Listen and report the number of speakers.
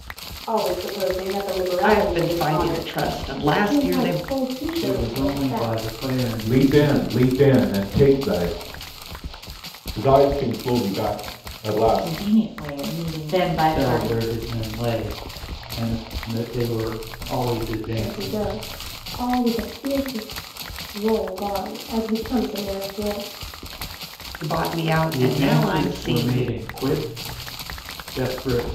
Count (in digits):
7